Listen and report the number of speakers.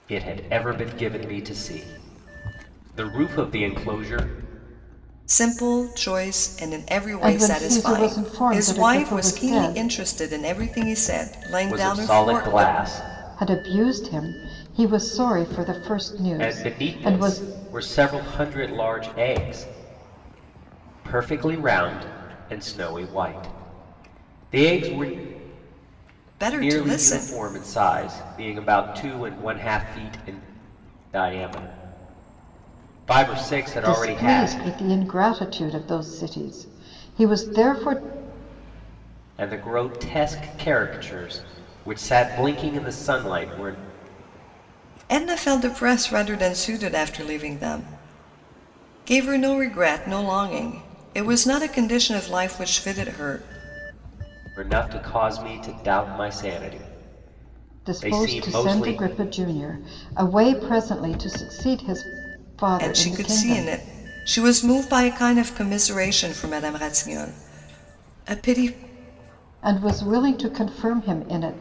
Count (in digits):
3